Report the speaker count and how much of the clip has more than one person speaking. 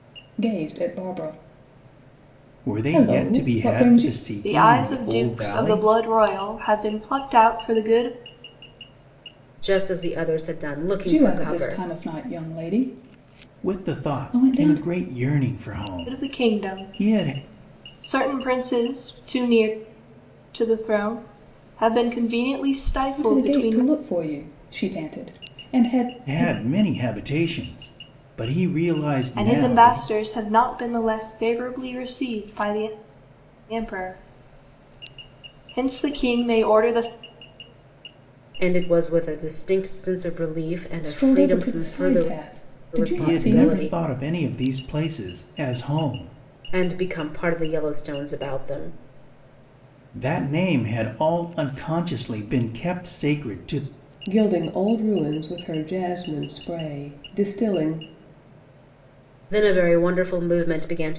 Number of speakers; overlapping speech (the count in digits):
4, about 17%